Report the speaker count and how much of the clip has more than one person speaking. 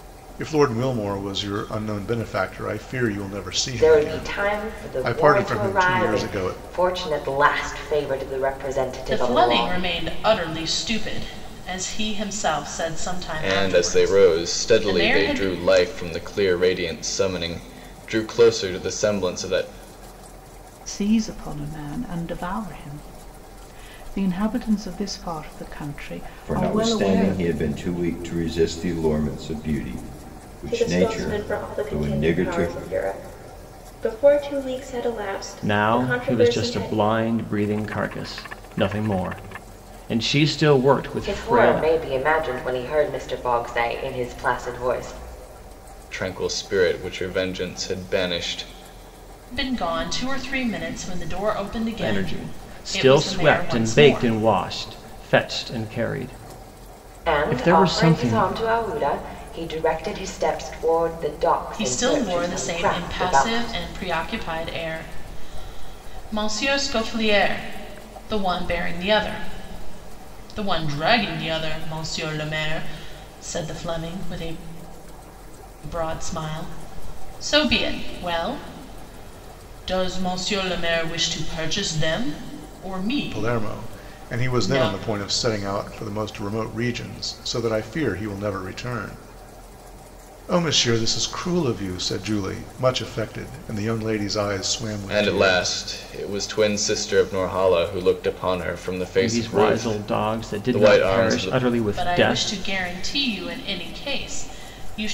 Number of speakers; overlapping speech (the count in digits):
8, about 21%